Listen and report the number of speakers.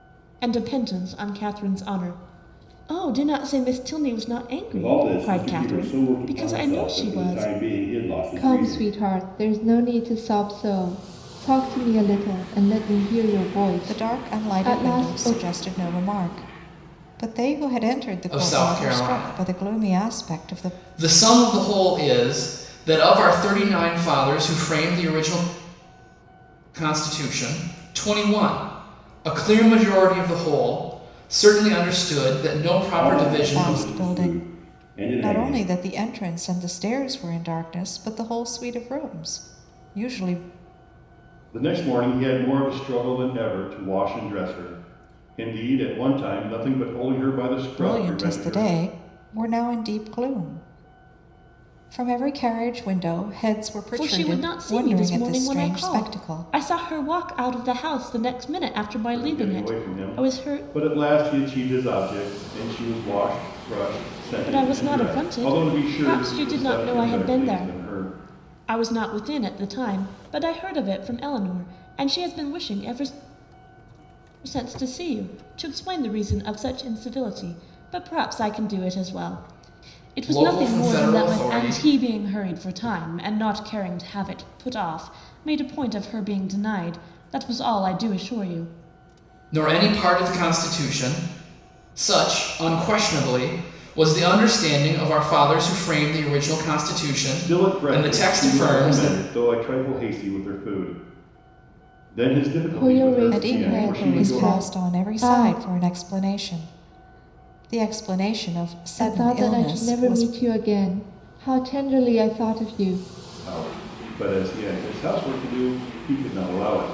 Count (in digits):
5